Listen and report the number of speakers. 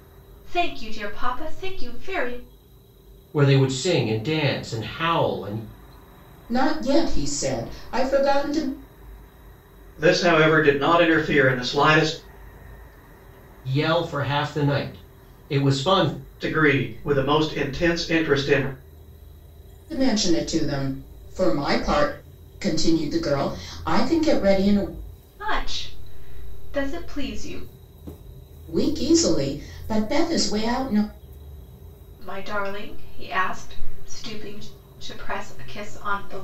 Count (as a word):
four